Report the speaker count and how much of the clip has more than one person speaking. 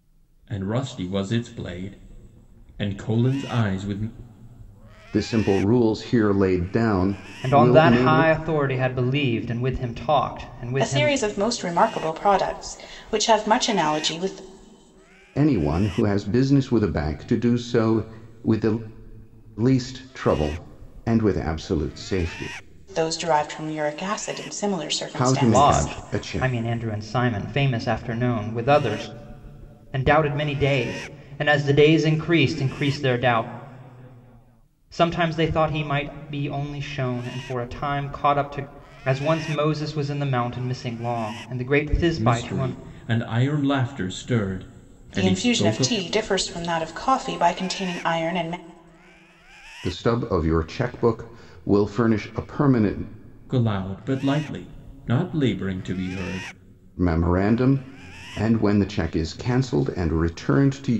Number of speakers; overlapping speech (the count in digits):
4, about 7%